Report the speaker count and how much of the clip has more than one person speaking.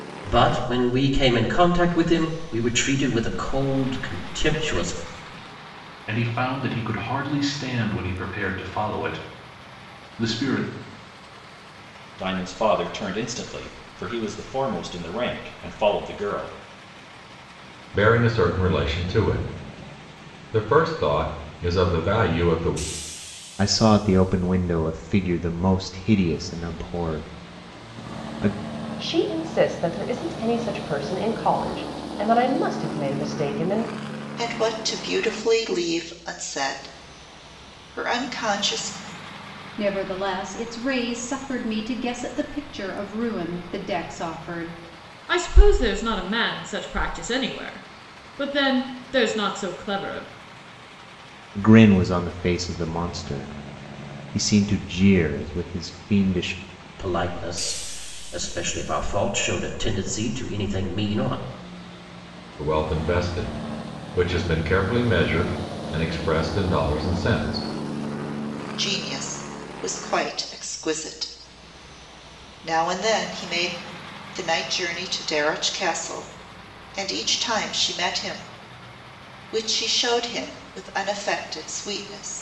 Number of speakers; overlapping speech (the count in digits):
9, no overlap